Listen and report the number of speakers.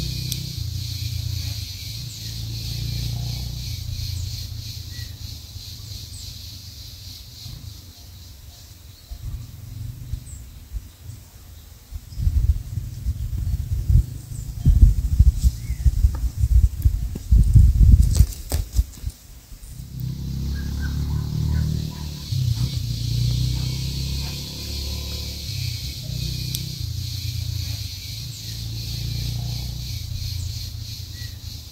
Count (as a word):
zero